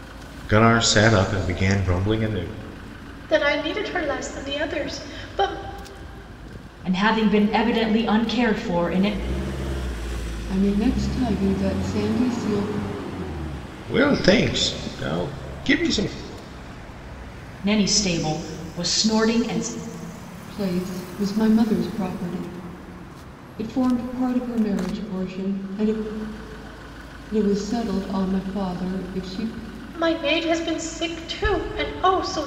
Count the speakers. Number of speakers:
4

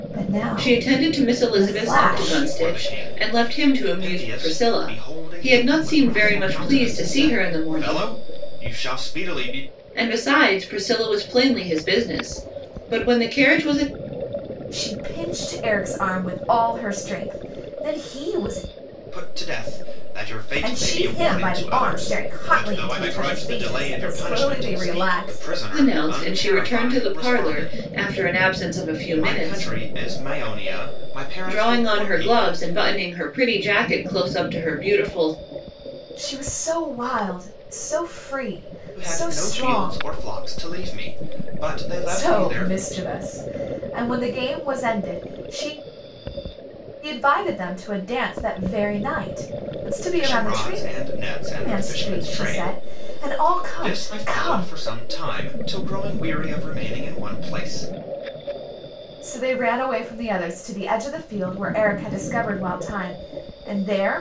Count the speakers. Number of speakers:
3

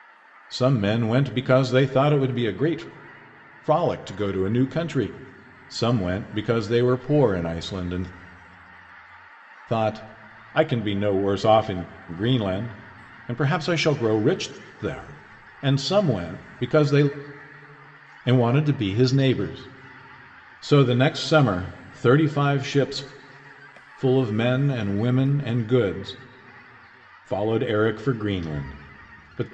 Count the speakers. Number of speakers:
1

